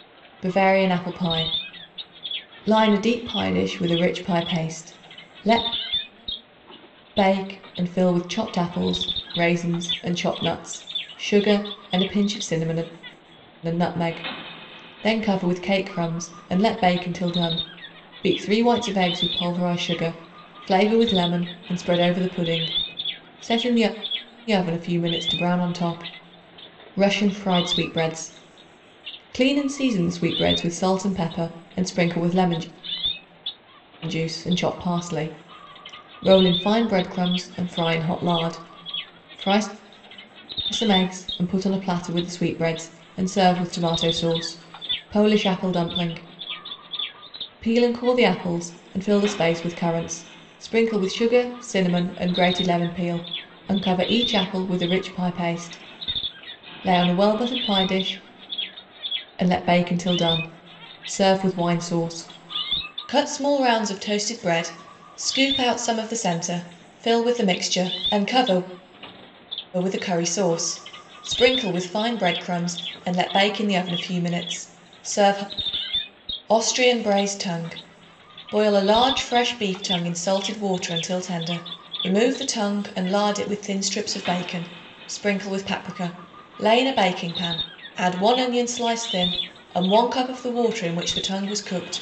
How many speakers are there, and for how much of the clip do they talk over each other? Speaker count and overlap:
1, no overlap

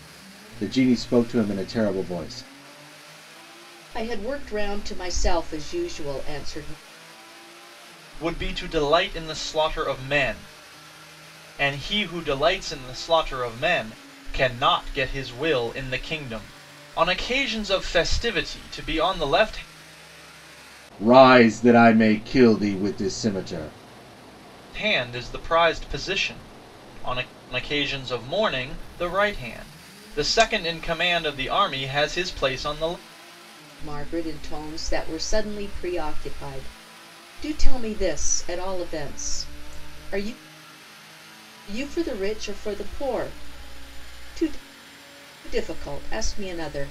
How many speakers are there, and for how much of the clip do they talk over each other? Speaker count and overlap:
3, no overlap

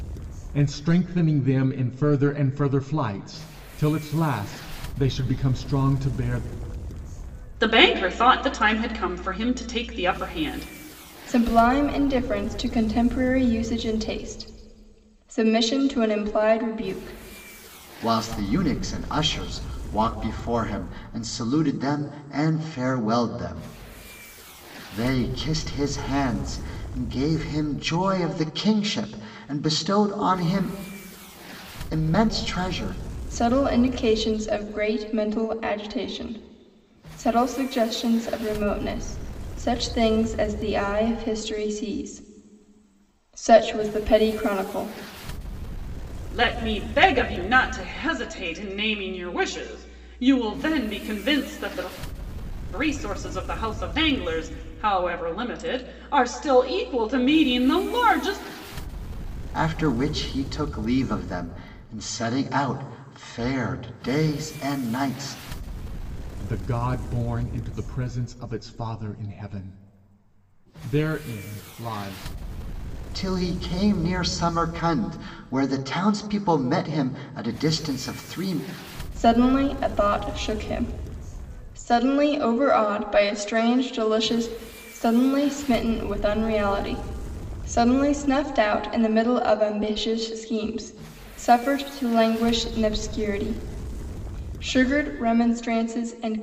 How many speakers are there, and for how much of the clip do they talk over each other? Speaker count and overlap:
4, no overlap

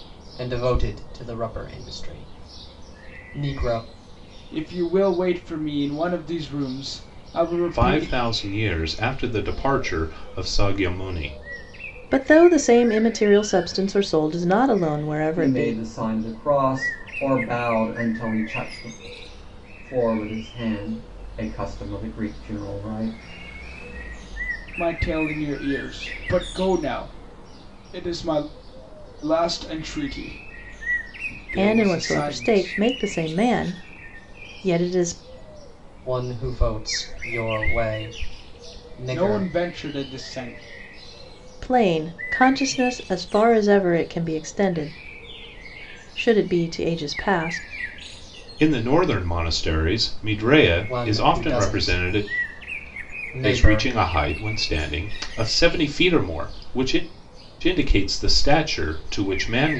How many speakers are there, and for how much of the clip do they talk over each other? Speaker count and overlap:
5, about 7%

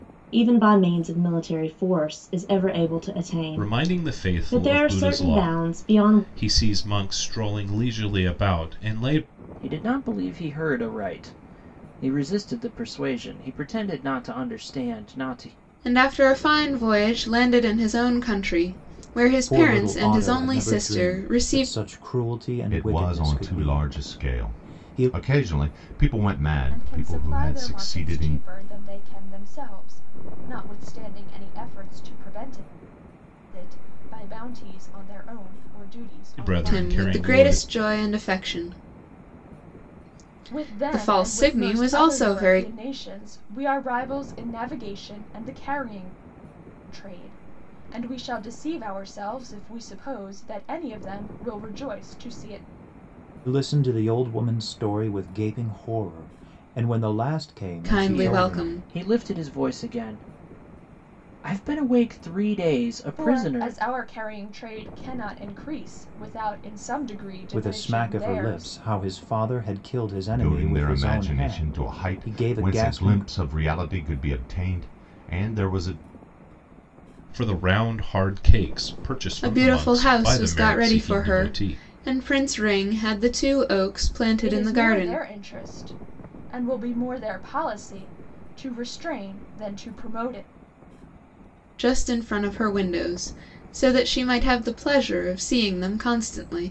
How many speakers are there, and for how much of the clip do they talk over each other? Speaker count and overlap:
7, about 23%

